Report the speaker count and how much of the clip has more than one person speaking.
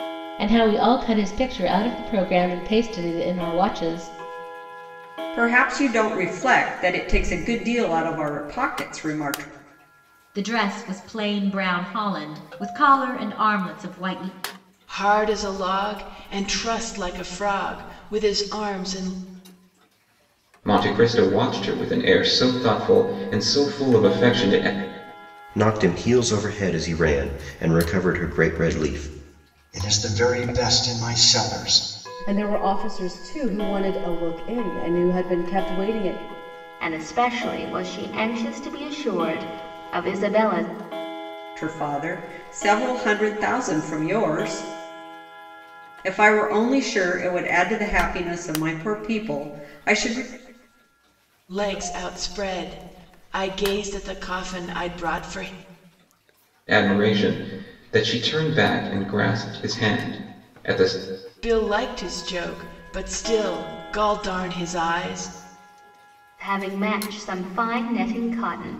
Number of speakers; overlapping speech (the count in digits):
9, no overlap